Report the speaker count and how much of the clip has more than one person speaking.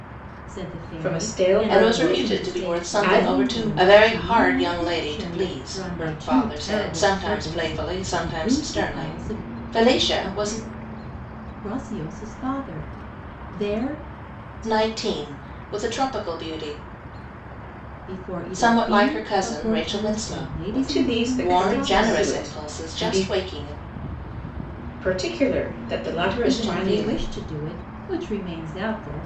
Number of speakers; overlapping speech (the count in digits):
3, about 49%